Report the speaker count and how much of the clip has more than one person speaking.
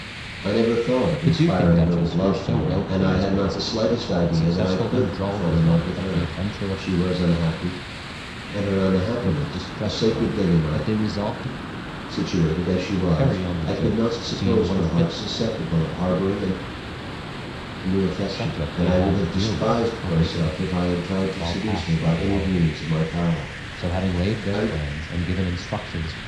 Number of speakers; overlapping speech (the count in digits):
2, about 50%